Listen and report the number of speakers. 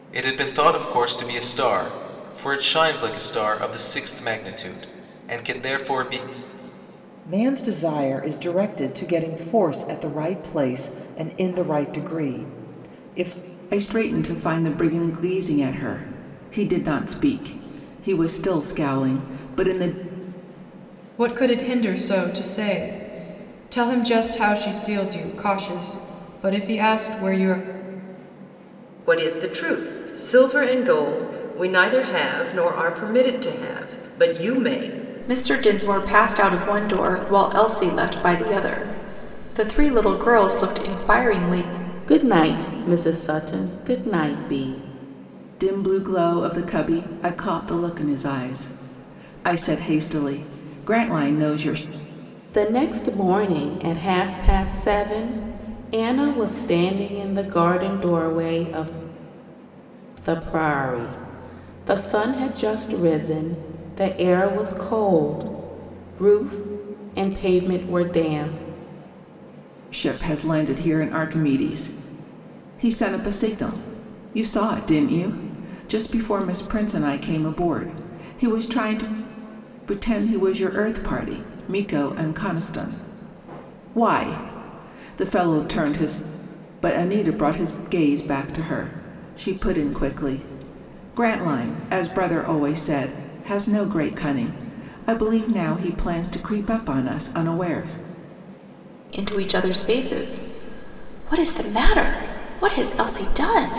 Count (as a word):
seven